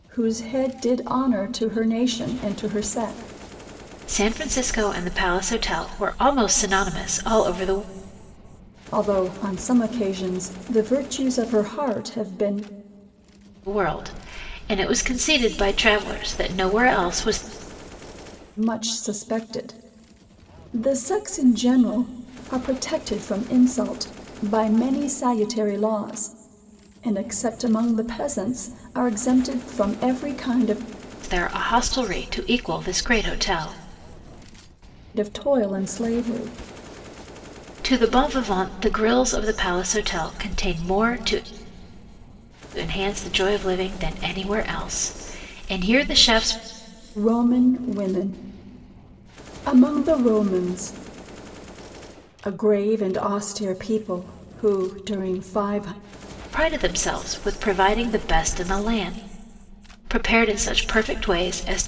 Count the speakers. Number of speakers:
2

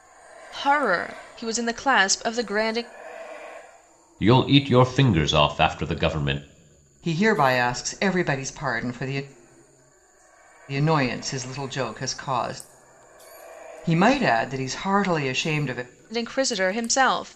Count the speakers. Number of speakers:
3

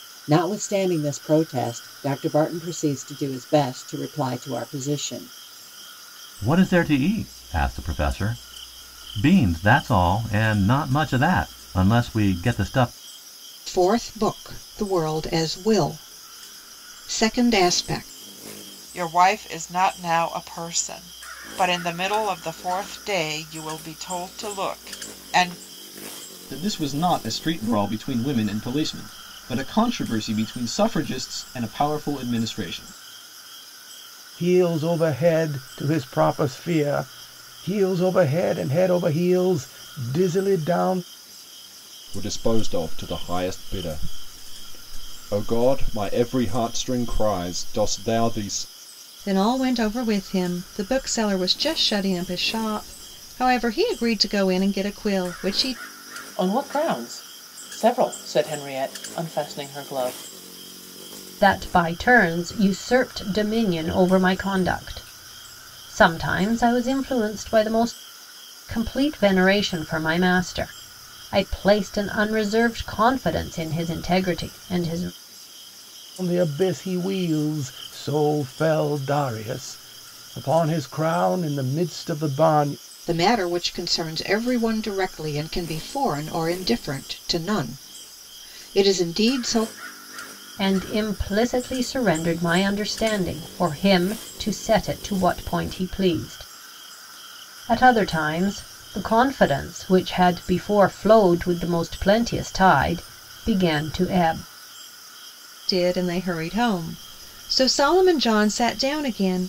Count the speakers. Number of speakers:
10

